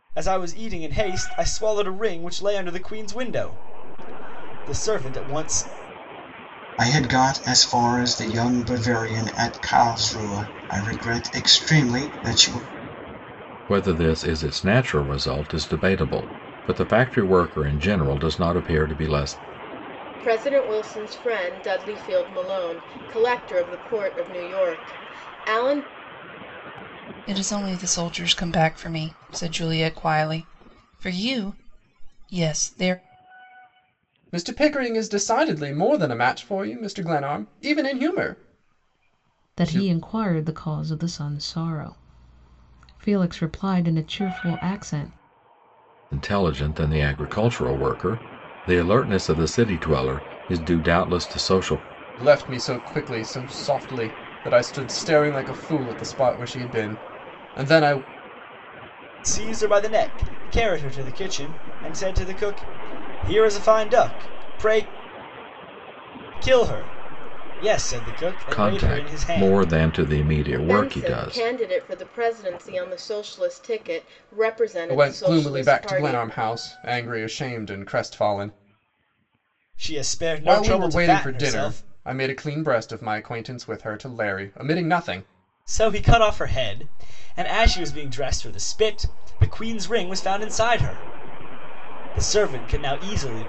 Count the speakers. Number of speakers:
seven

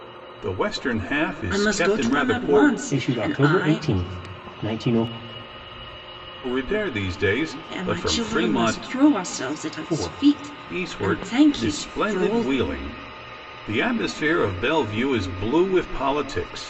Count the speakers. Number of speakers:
three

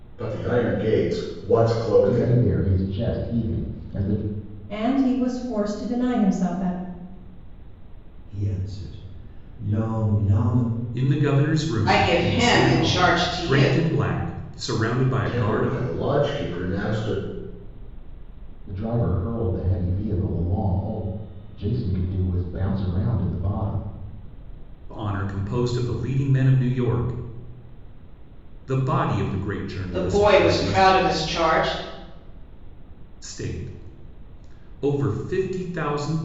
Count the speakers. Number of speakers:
six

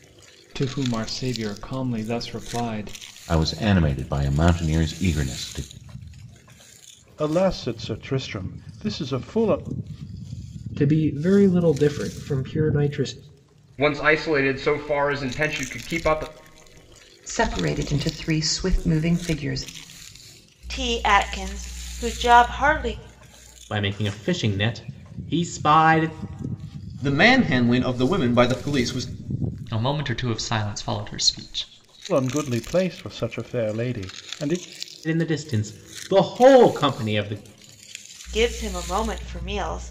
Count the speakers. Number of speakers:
ten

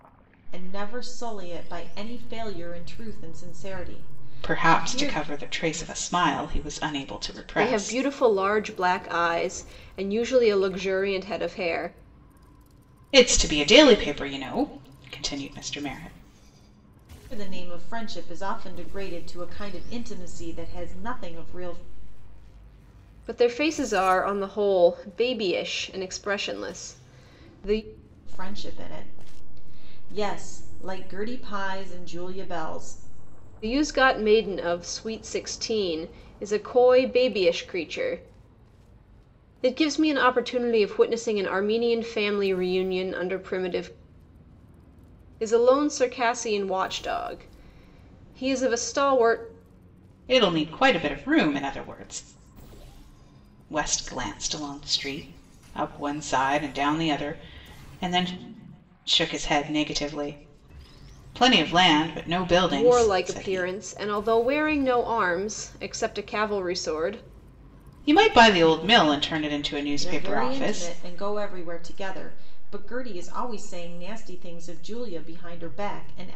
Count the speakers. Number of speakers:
three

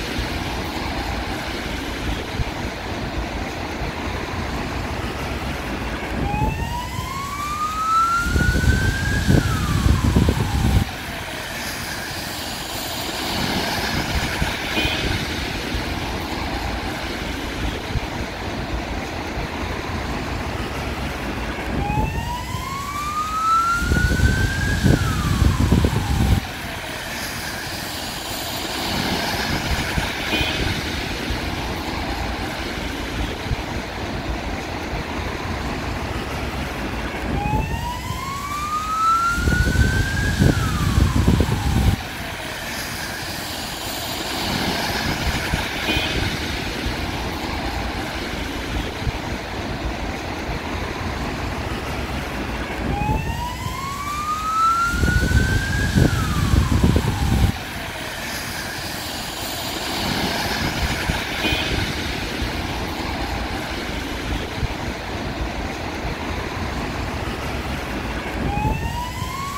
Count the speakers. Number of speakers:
zero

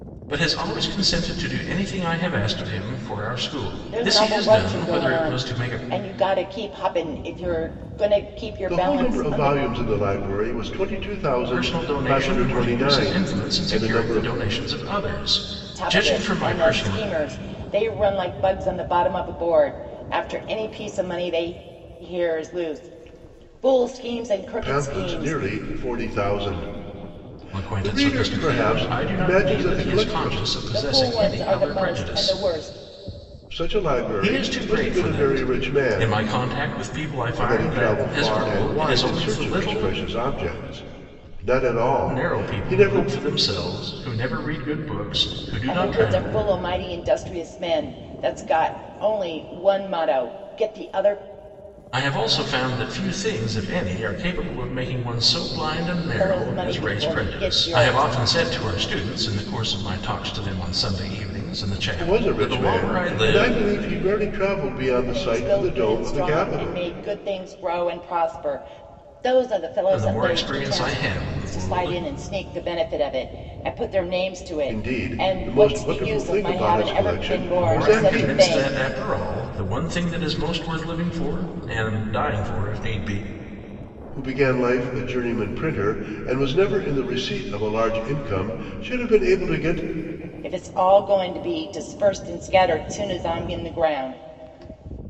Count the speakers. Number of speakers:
three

